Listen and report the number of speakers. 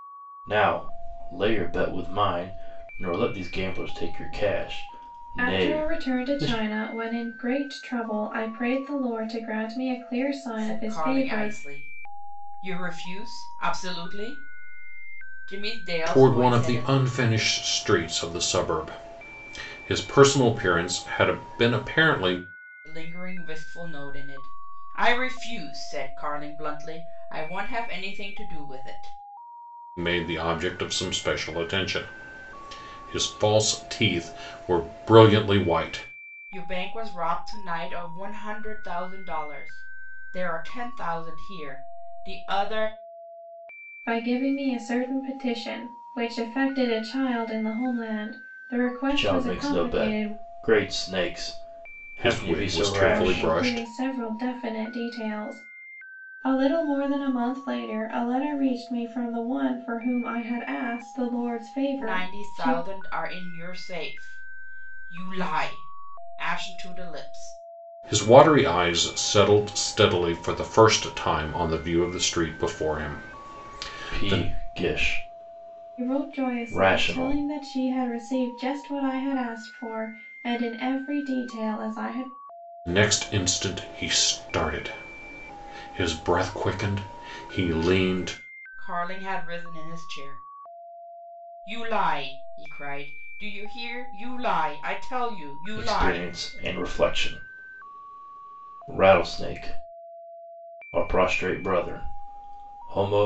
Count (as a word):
four